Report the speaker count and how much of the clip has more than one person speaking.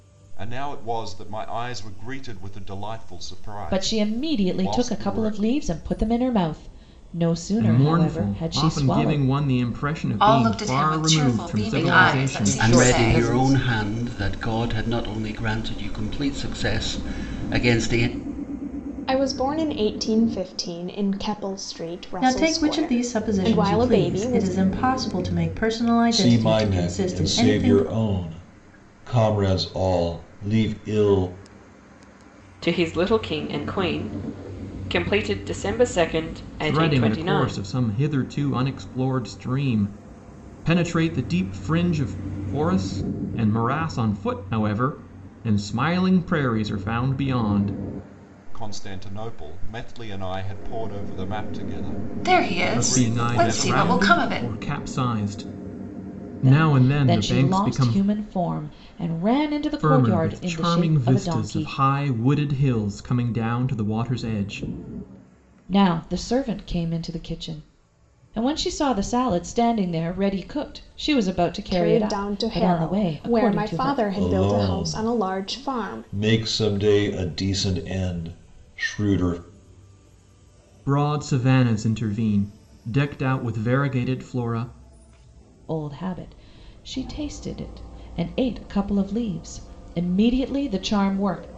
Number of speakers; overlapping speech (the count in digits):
10, about 25%